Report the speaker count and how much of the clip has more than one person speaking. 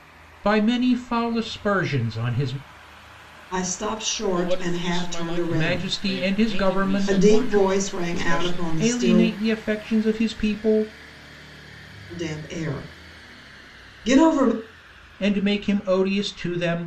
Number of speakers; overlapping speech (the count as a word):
three, about 30%